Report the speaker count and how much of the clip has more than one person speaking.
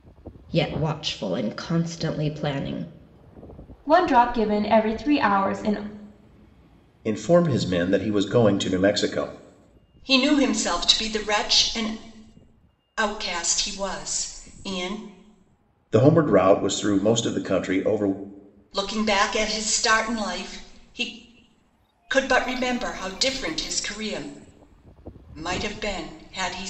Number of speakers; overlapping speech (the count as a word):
four, no overlap